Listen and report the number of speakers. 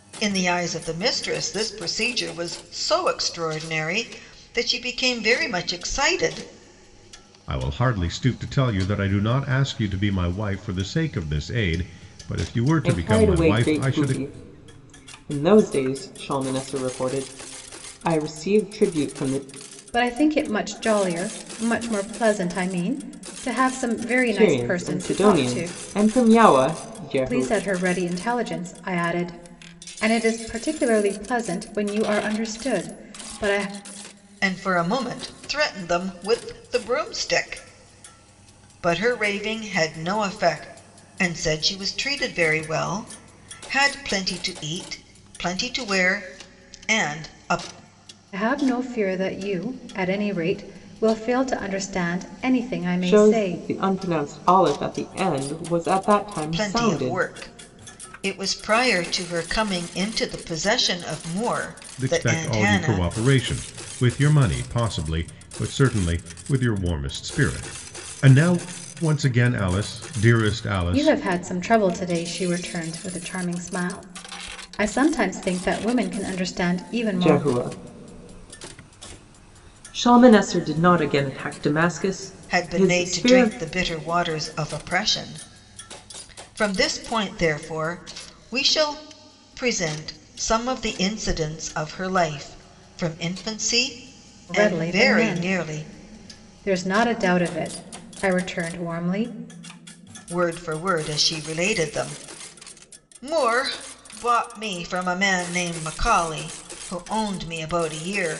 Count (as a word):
four